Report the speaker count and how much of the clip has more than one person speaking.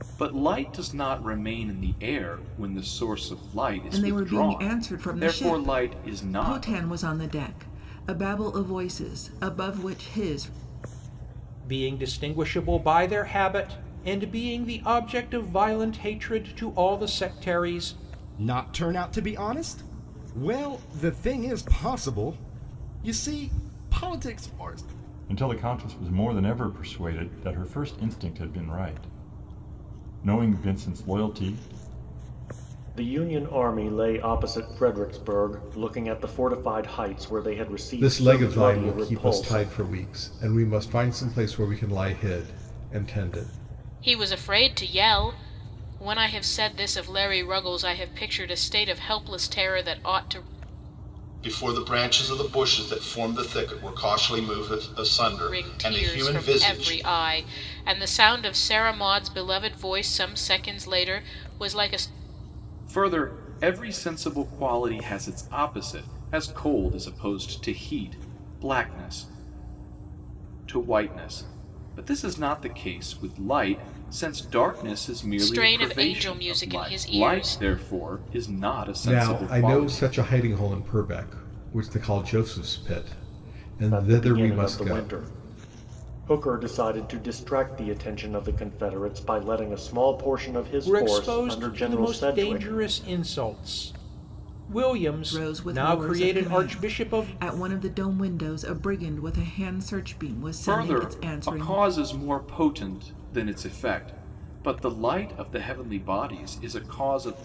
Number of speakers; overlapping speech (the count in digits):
9, about 15%